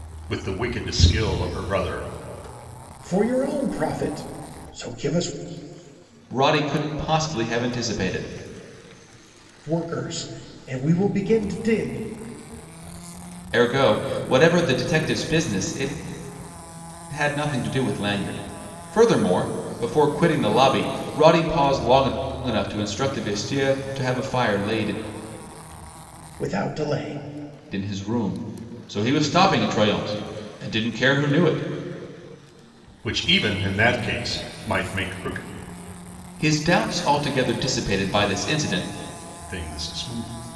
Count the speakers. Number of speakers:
3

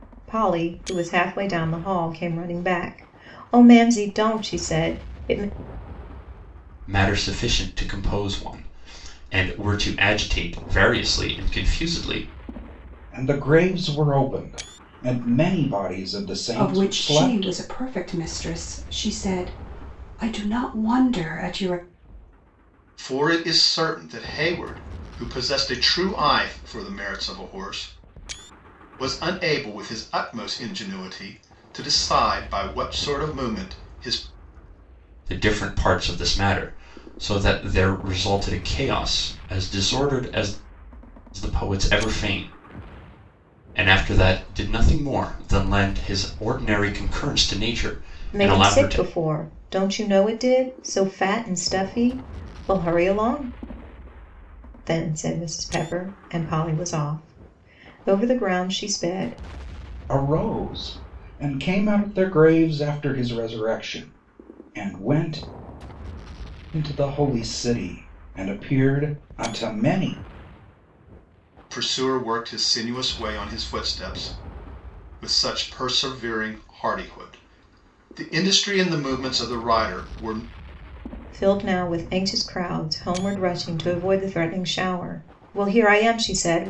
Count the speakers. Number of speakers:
5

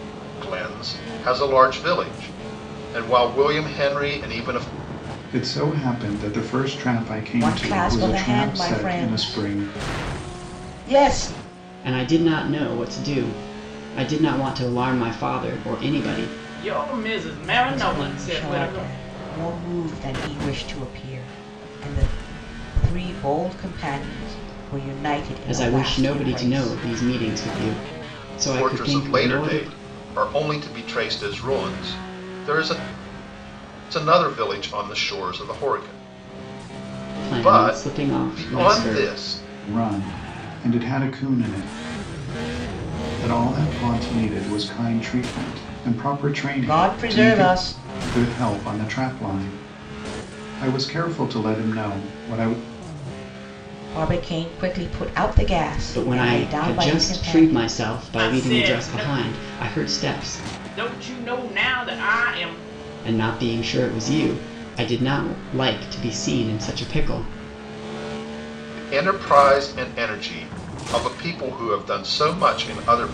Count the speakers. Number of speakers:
5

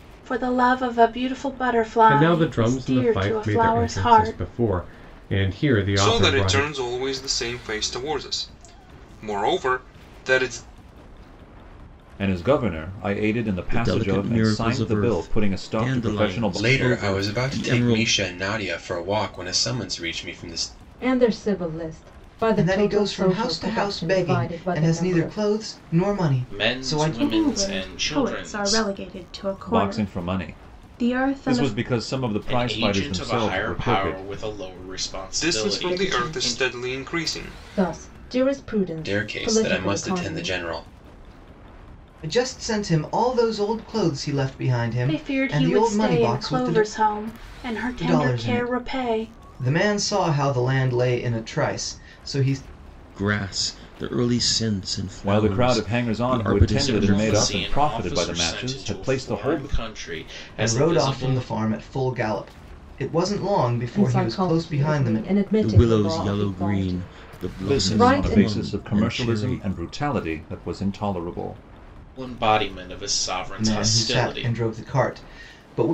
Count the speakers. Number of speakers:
10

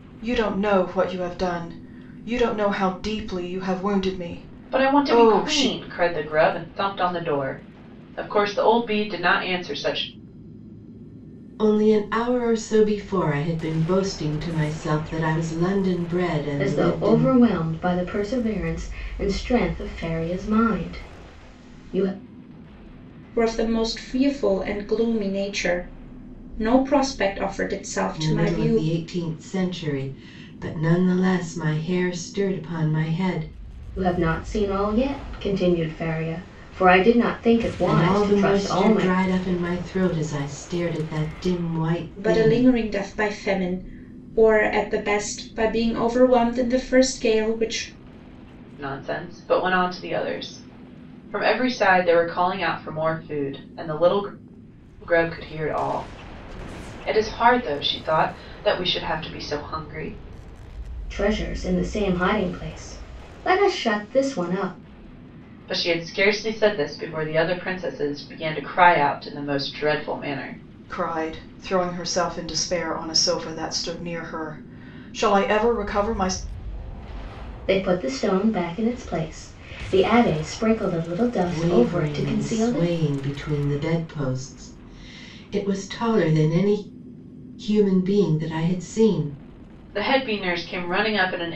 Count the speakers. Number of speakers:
5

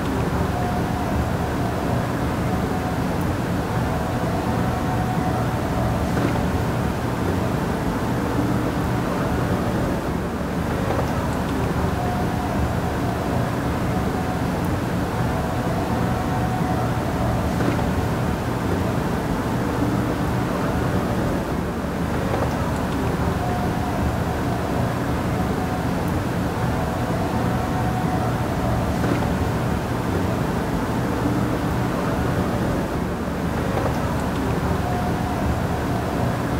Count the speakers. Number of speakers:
0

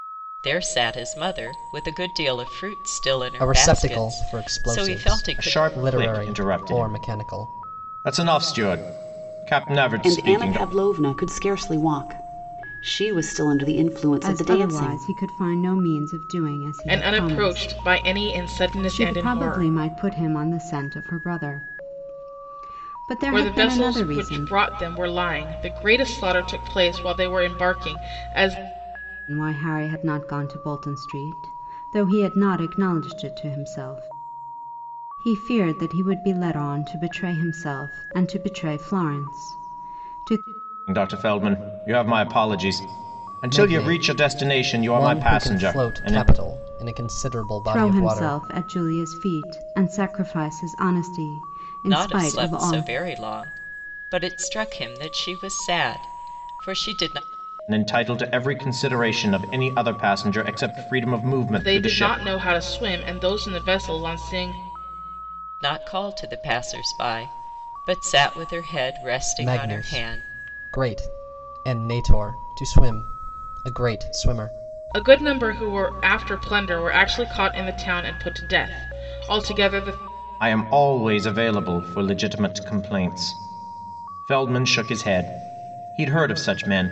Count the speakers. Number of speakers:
6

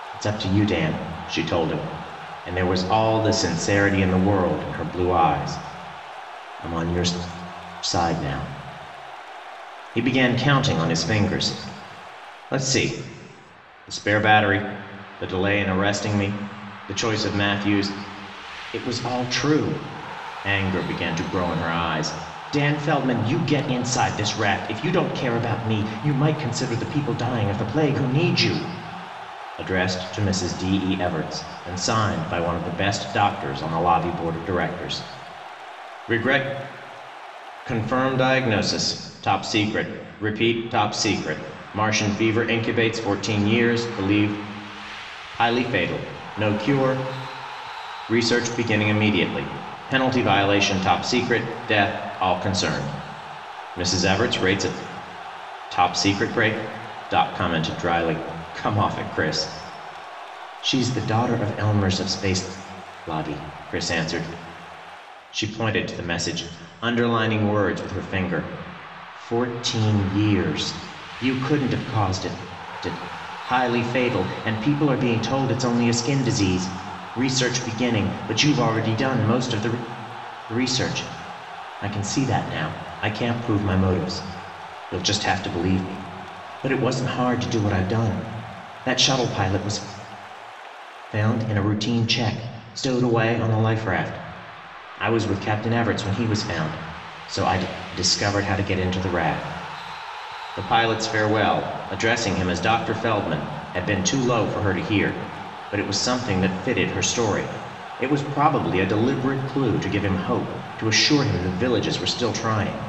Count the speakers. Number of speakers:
1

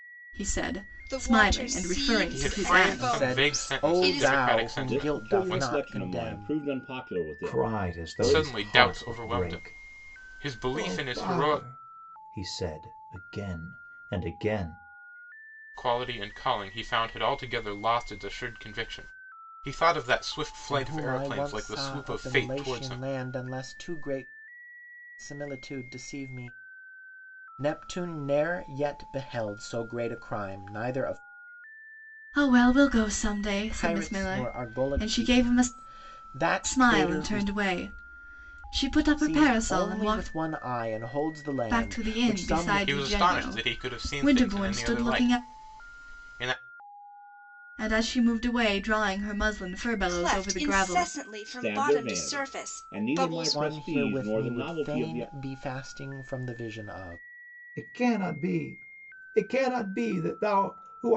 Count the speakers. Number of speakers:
6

